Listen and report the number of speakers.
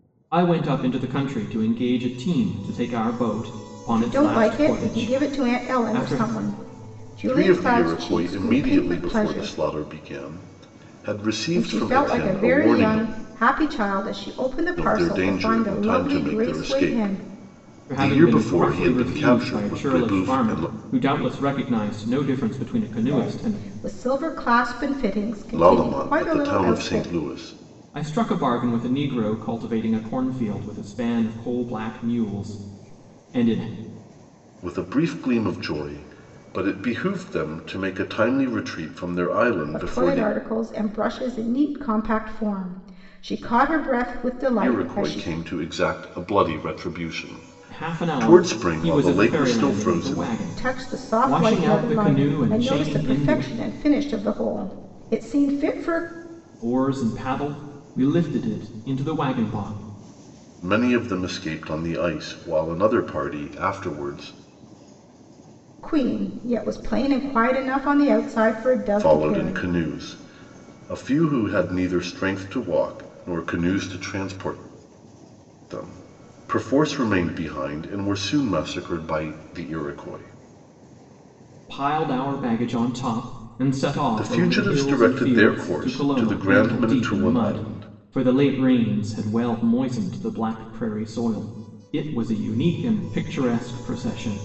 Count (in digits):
3